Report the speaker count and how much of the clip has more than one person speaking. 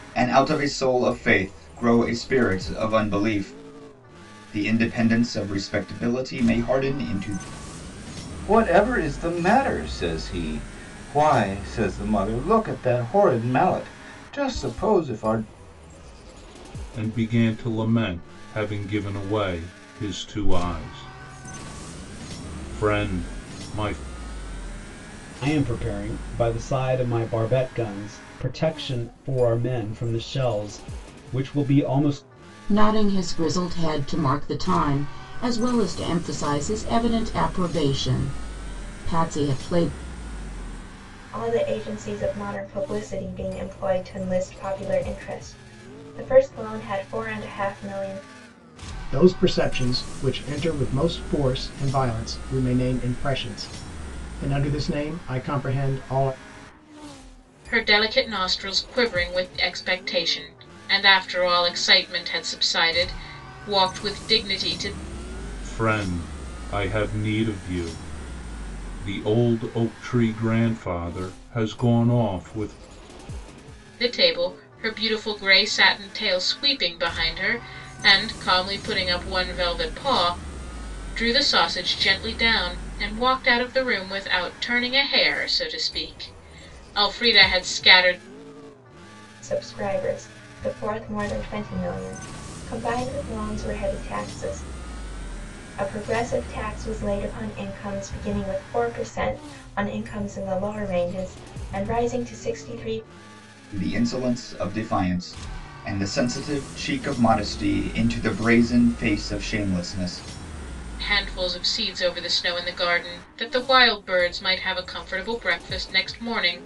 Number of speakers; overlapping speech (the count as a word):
eight, no overlap